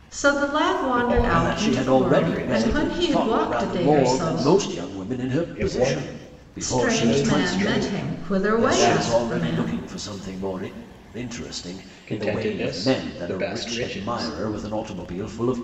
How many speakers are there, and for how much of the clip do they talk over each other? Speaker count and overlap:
3, about 68%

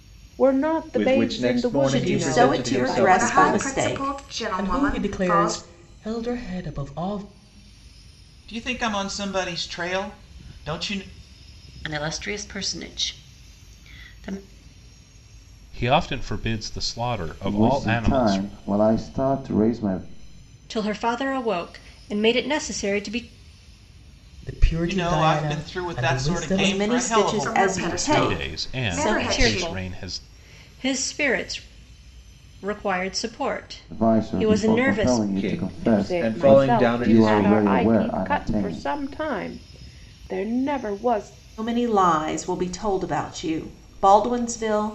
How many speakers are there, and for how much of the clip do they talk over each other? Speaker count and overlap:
10, about 35%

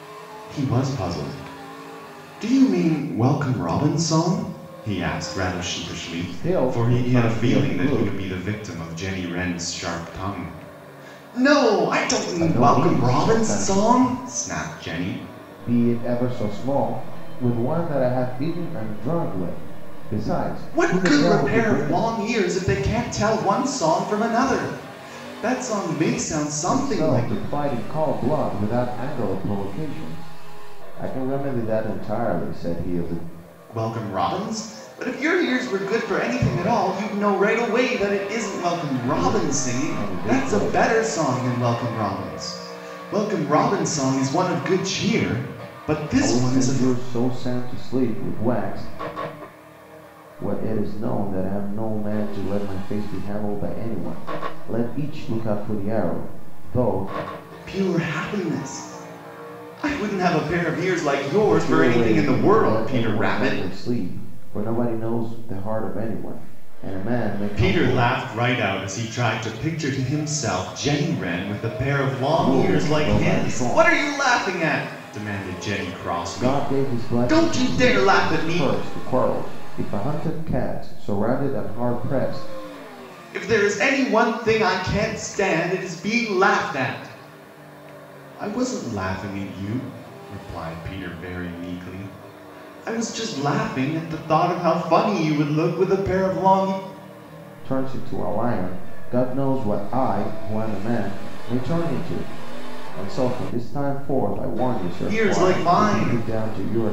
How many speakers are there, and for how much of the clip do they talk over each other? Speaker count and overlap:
2, about 15%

